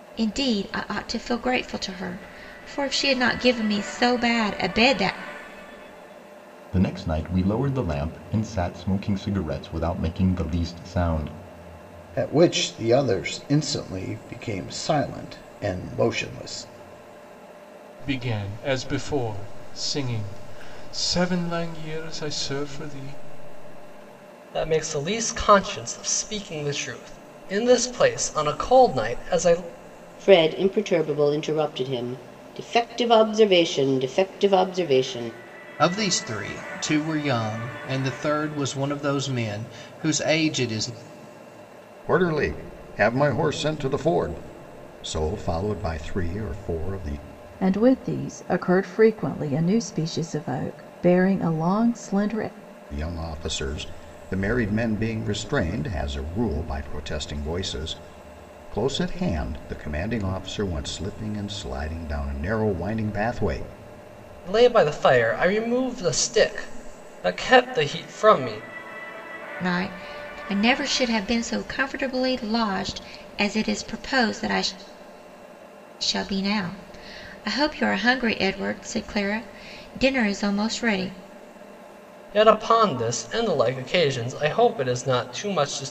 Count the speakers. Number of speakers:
9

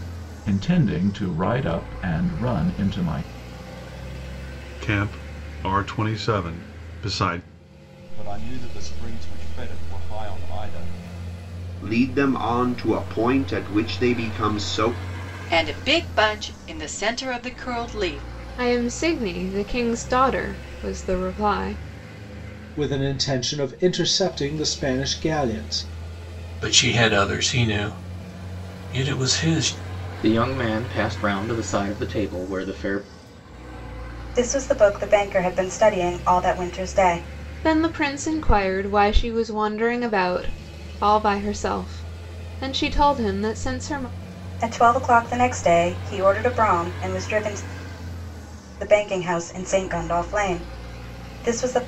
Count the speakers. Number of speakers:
10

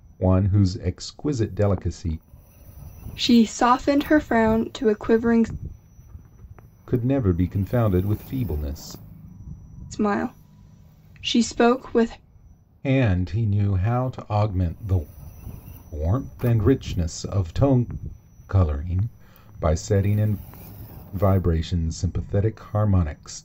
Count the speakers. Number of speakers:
2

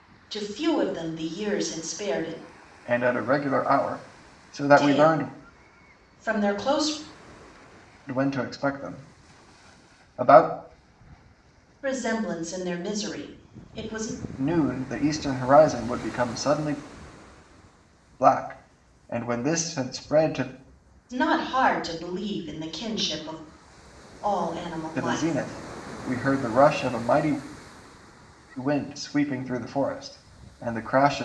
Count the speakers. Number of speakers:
2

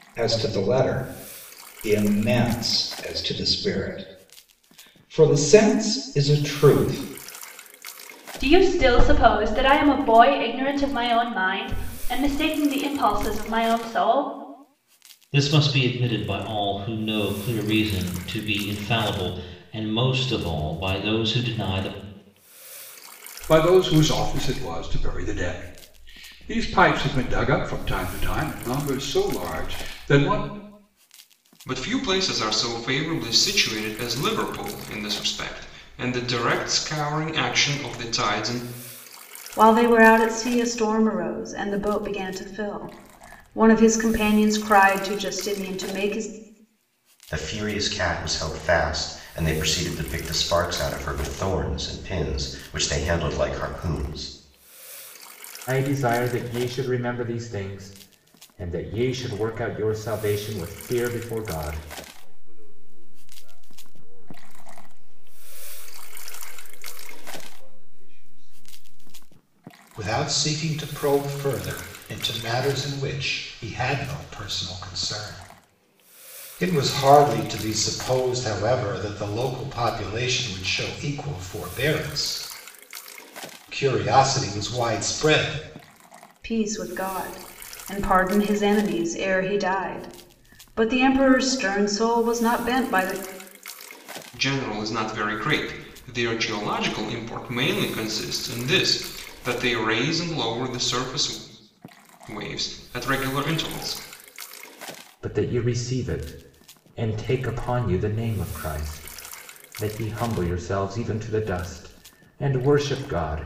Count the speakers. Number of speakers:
10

